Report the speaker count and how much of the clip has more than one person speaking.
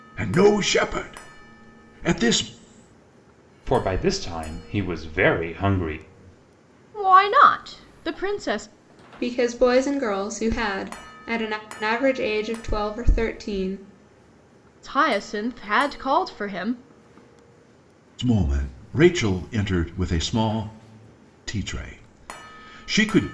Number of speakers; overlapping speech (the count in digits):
4, no overlap